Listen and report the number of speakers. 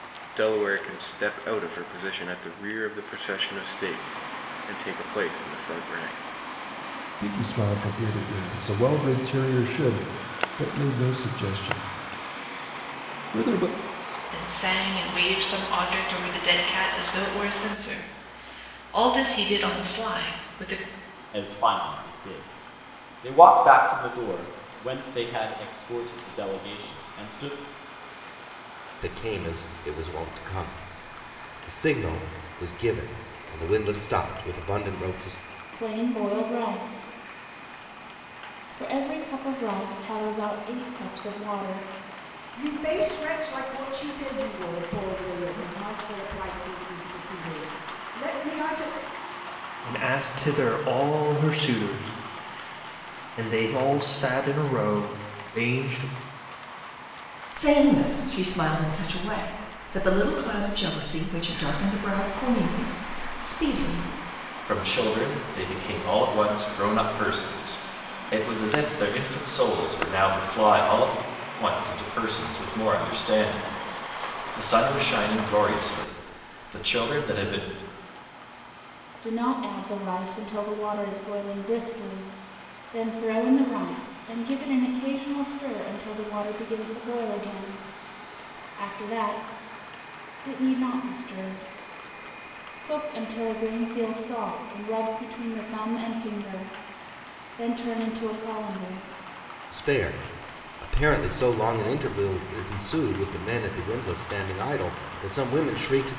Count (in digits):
10